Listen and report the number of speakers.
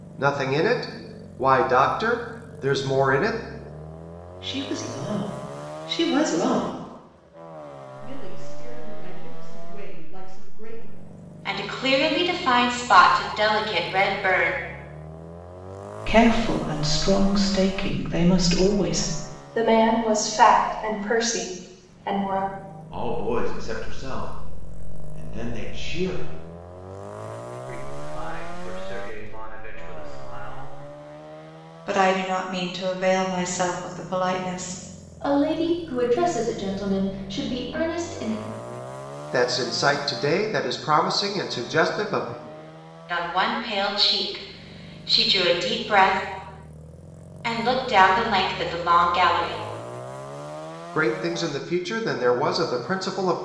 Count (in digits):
10